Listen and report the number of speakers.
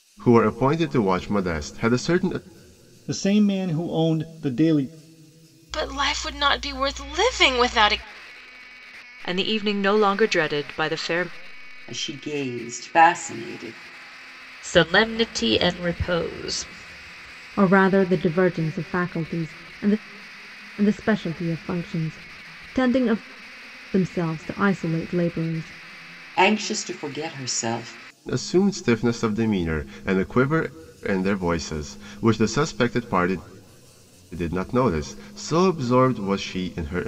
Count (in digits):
7